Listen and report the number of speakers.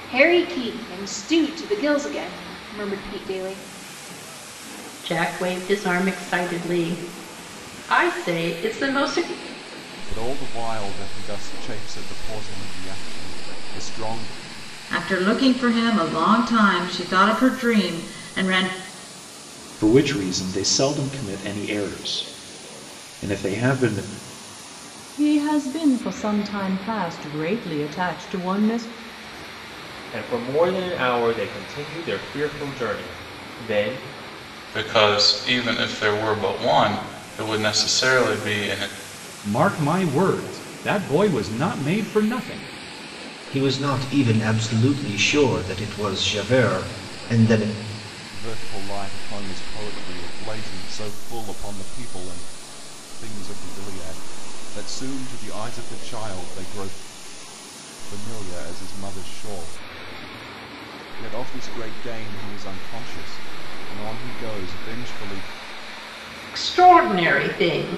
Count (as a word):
ten